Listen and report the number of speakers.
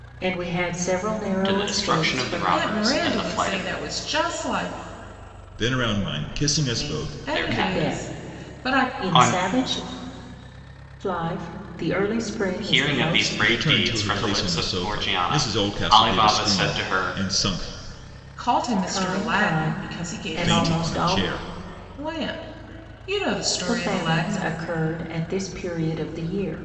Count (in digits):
4